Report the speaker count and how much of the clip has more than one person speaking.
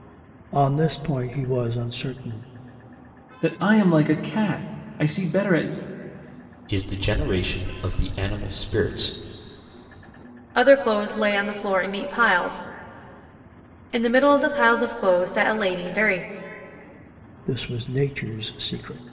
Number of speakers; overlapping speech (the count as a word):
four, no overlap